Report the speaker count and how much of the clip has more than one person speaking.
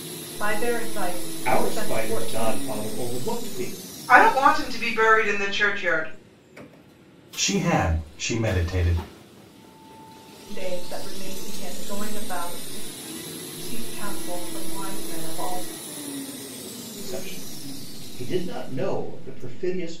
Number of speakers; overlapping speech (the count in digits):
4, about 6%